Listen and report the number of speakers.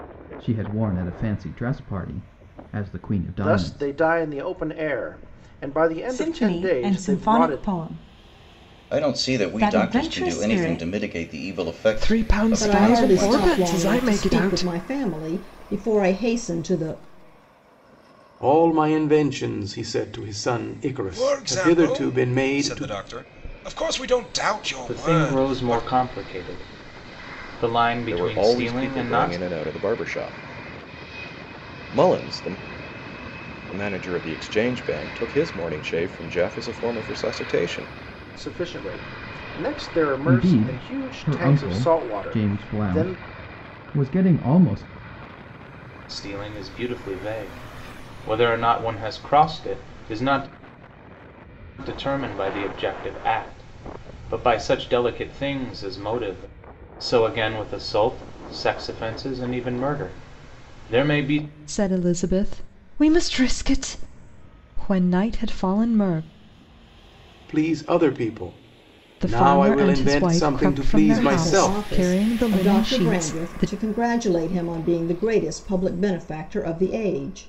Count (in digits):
10